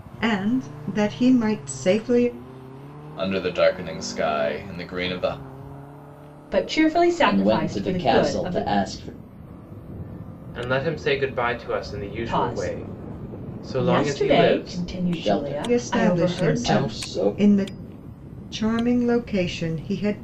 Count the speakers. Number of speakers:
five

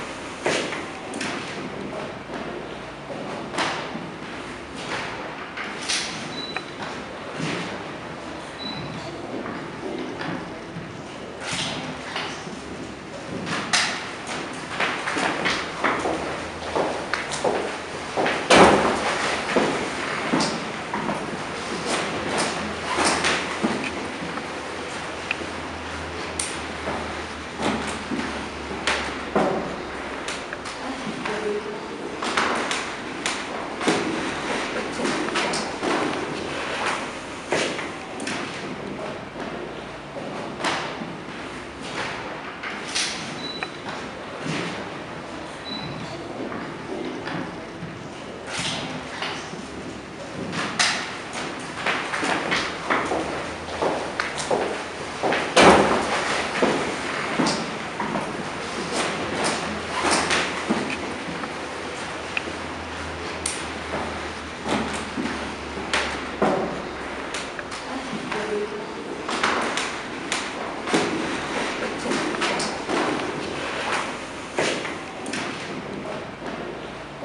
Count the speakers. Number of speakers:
zero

